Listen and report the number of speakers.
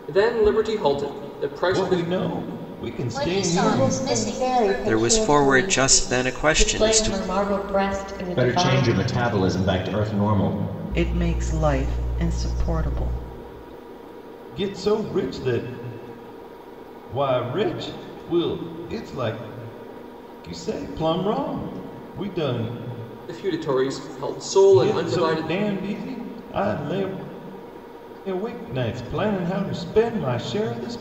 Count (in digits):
8